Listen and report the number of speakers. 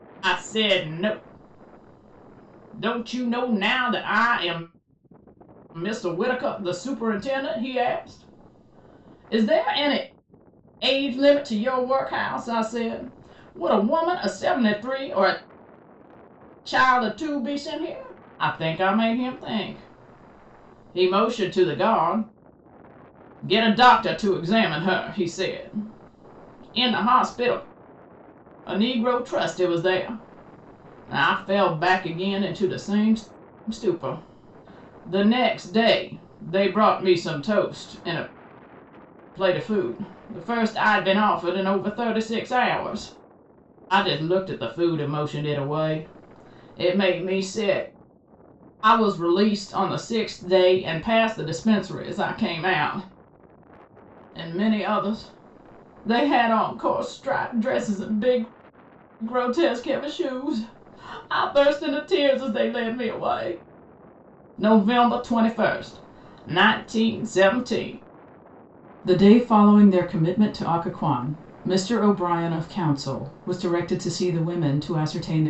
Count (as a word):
one